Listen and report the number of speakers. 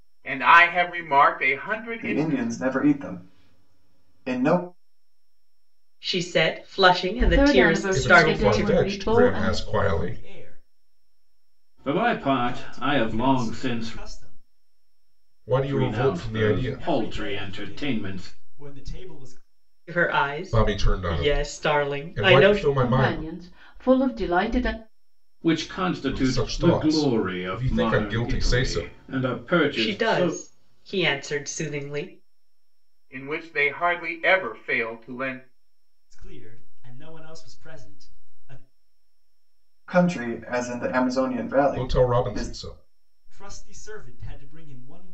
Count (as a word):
seven